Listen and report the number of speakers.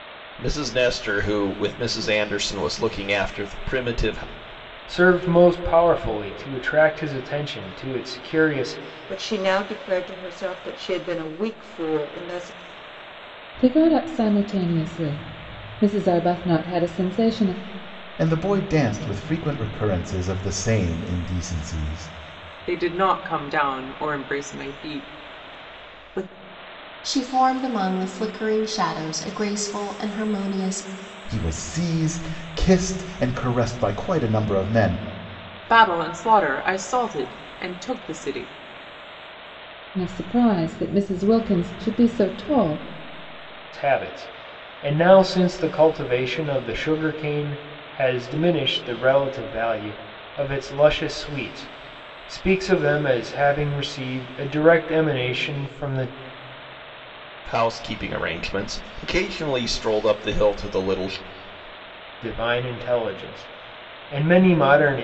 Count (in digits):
7